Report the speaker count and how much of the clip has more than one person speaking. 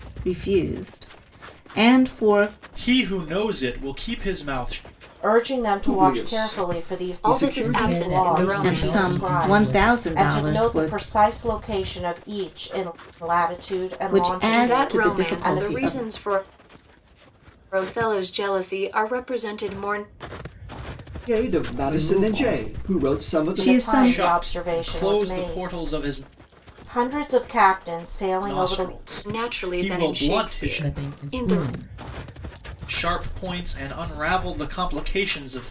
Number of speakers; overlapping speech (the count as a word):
six, about 39%